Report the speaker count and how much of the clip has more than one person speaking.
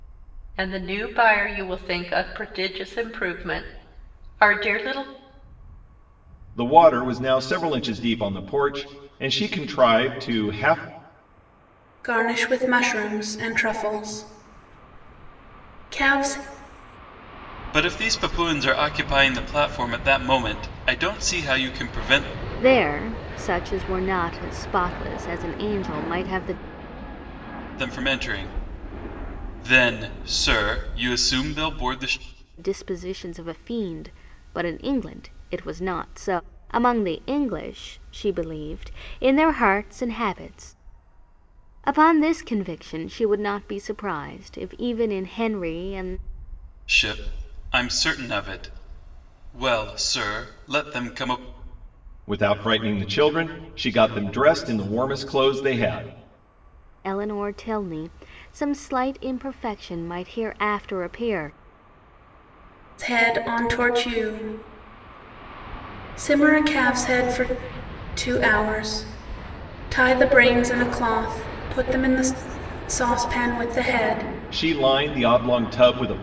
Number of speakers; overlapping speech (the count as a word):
five, no overlap